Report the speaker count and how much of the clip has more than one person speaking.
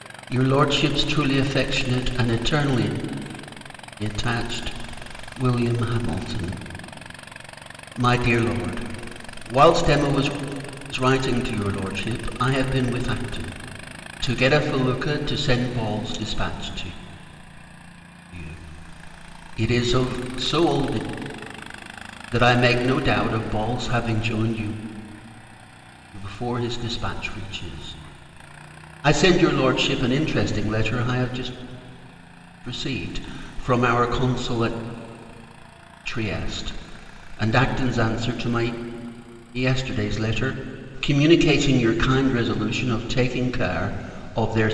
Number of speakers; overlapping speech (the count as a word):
one, no overlap